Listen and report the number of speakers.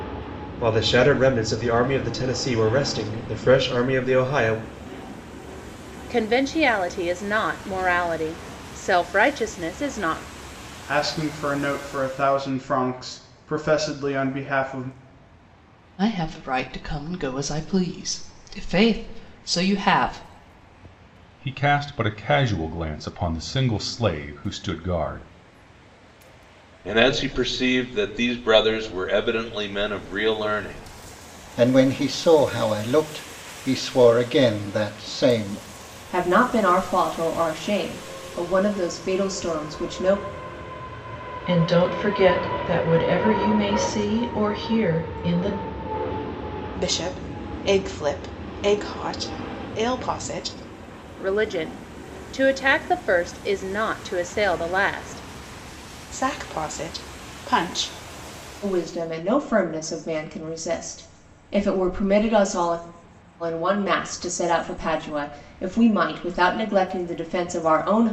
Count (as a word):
ten